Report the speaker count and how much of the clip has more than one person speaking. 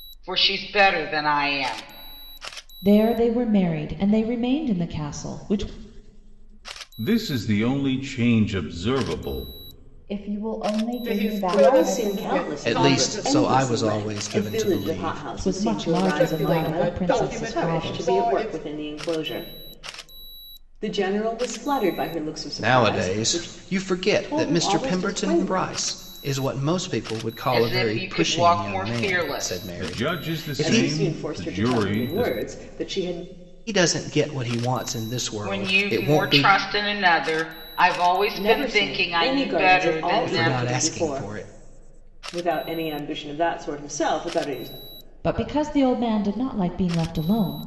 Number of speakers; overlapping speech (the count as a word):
seven, about 40%